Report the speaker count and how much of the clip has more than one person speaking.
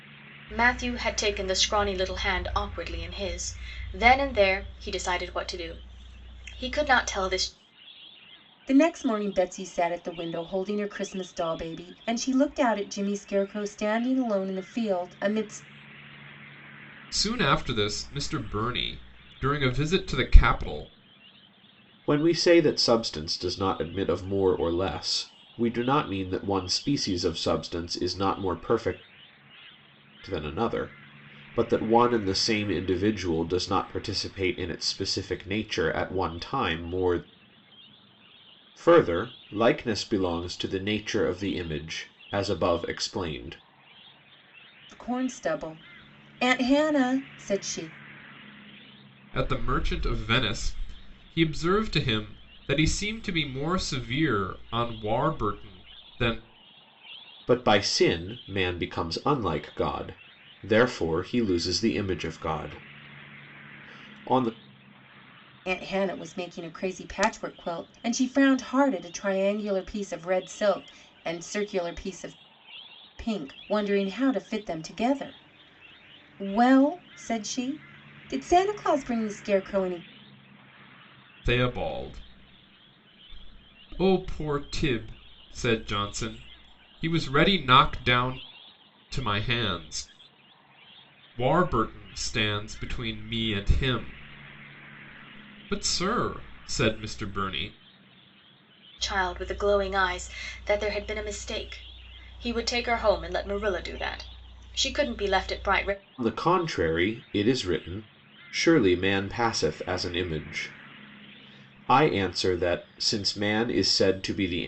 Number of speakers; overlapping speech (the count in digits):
4, no overlap